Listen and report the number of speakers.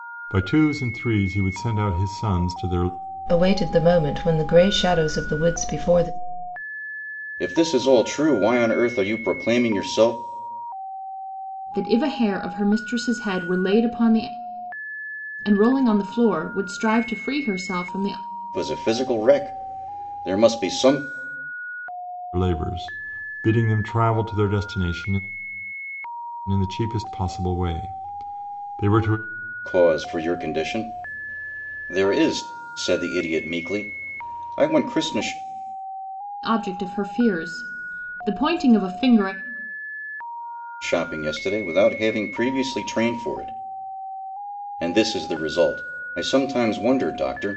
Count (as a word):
four